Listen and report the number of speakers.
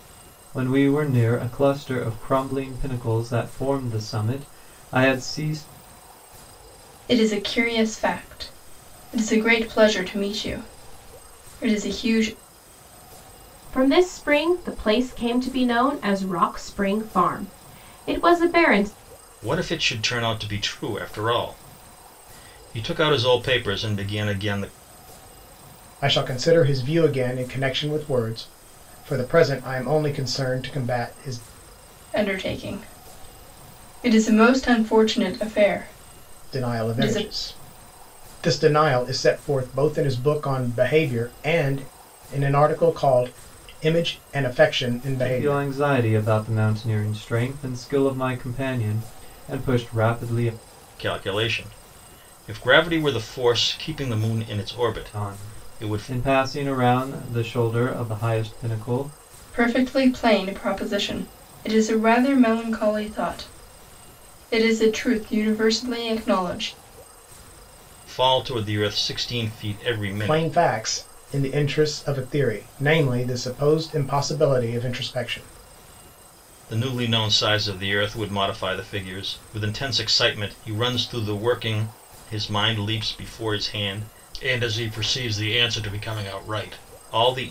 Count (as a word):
five